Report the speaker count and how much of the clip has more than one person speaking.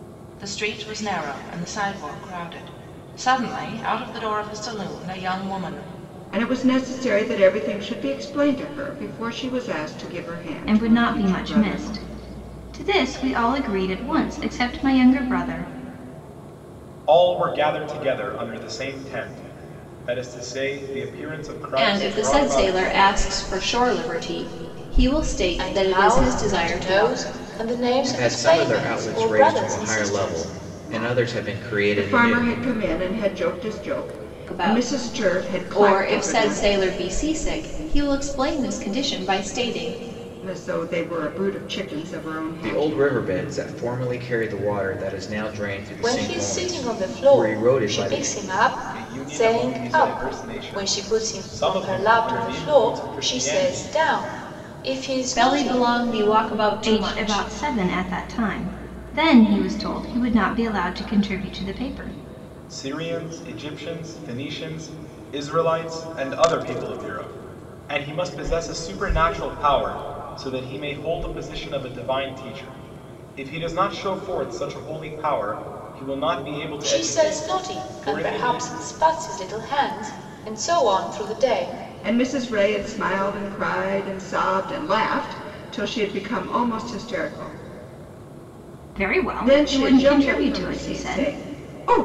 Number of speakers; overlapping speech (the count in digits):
7, about 25%